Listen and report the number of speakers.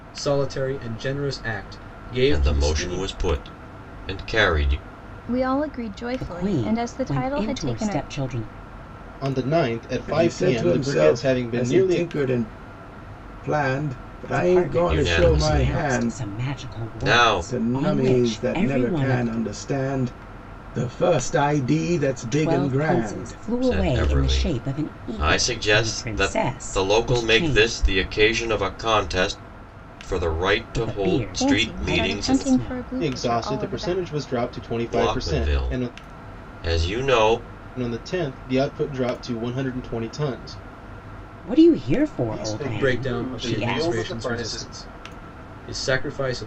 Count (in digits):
6